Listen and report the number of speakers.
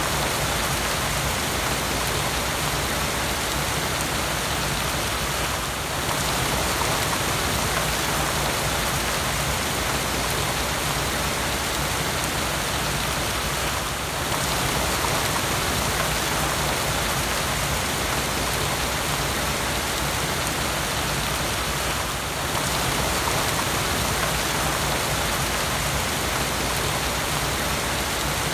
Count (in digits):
0